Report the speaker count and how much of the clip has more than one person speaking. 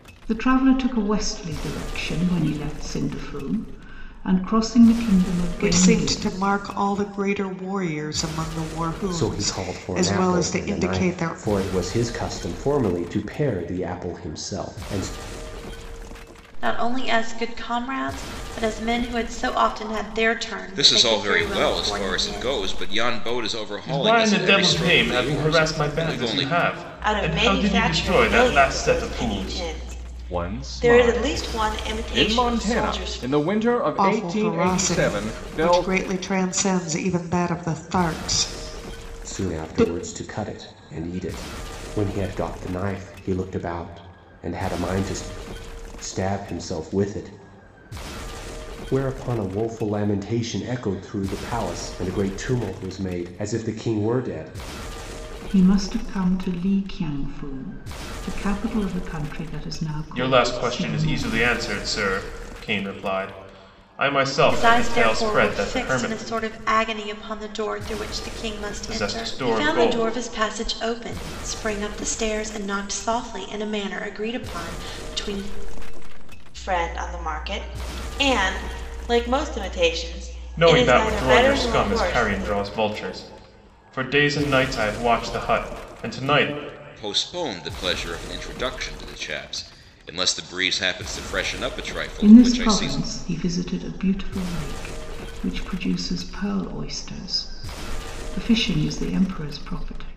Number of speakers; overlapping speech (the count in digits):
8, about 23%